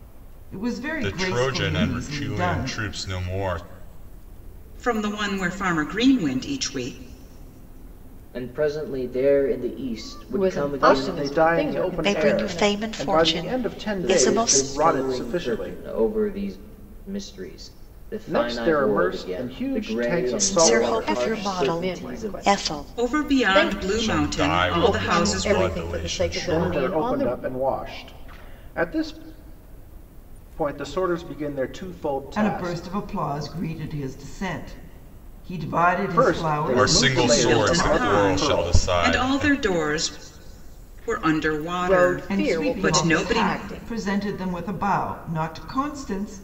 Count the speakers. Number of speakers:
seven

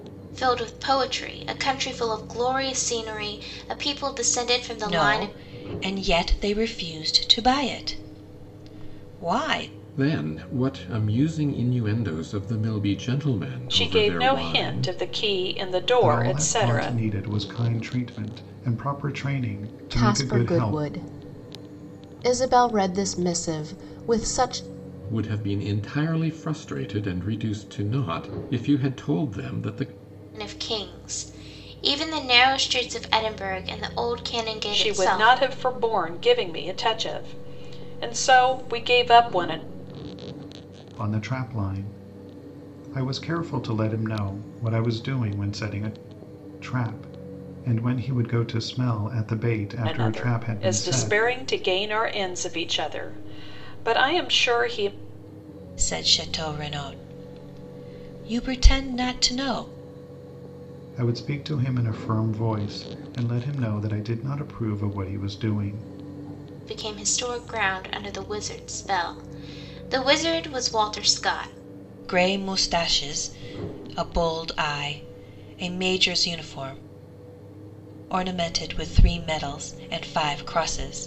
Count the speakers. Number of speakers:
six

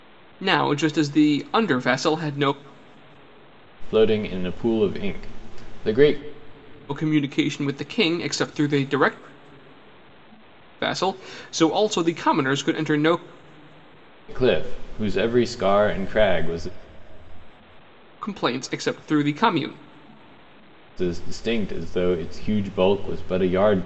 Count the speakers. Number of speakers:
two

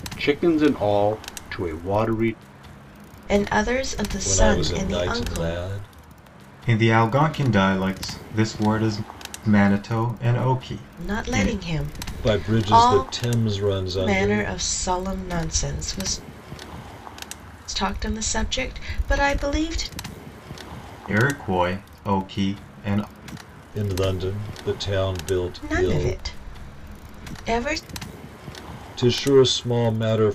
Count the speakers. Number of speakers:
four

